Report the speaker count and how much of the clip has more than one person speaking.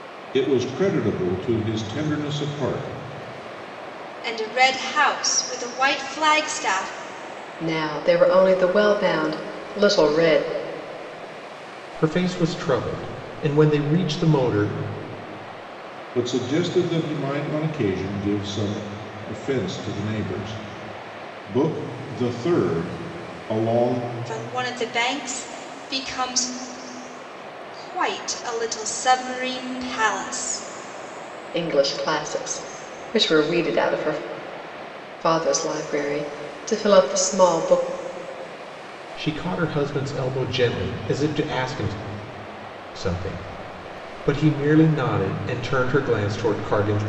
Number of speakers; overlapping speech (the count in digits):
4, no overlap